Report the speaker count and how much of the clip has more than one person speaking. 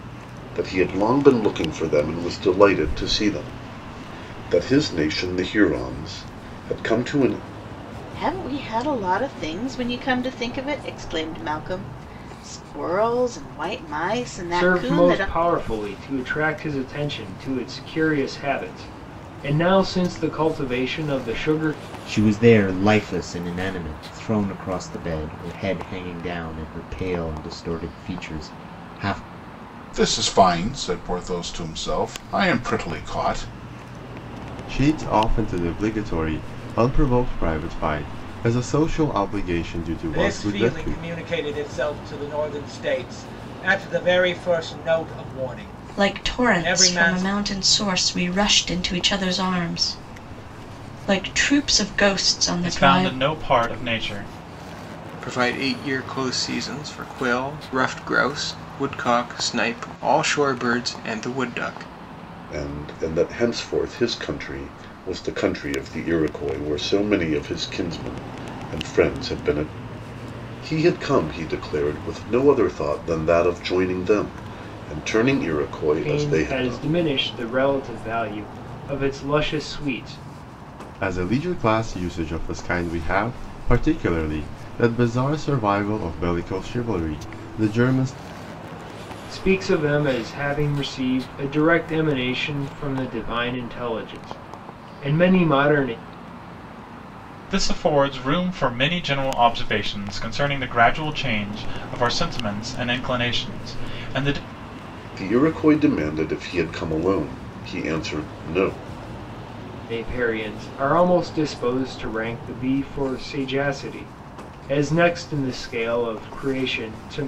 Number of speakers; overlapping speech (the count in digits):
10, about 4%